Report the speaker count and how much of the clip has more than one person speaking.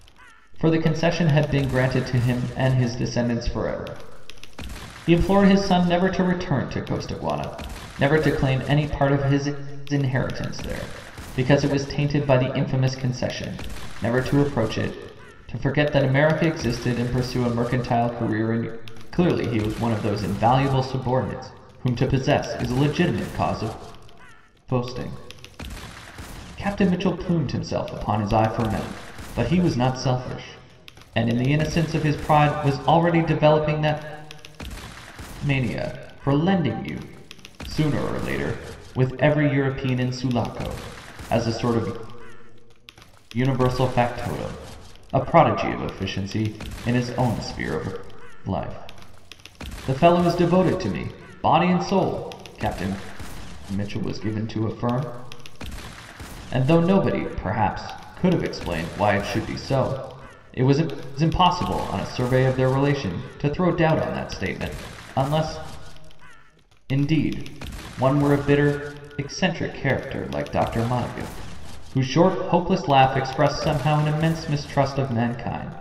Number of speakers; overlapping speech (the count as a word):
one, no overlap